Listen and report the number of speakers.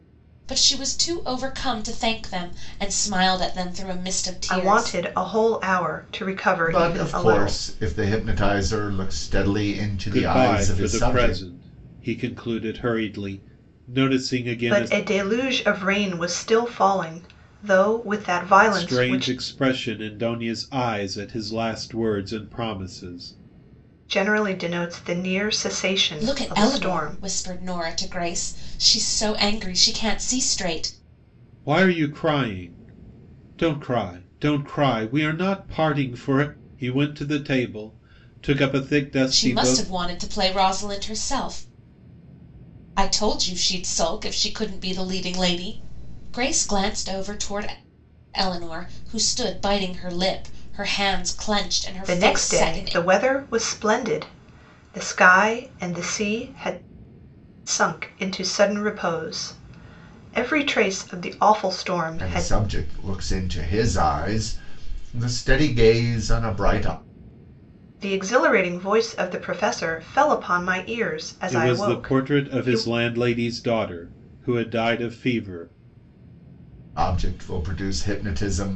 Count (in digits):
4